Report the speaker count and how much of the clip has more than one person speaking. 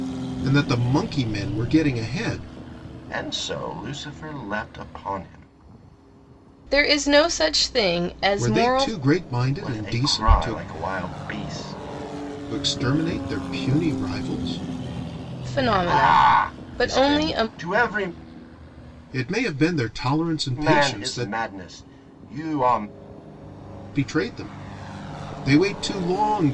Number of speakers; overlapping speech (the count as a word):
three, about 16%